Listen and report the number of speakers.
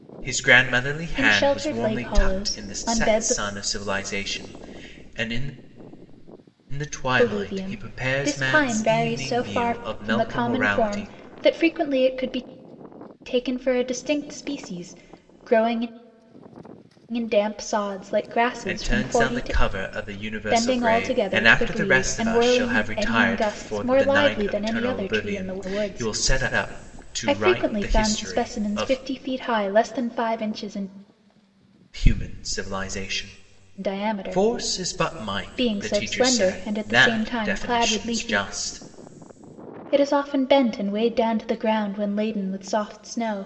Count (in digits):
2